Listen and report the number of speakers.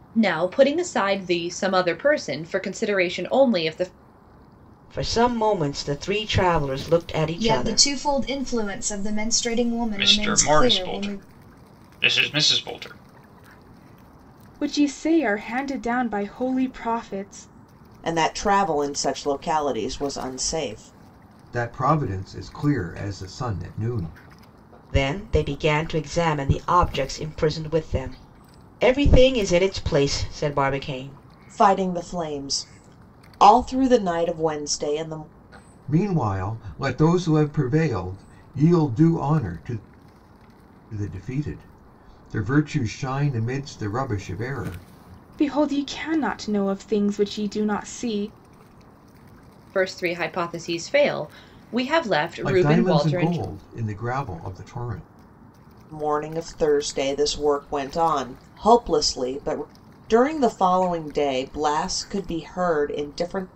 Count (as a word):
seven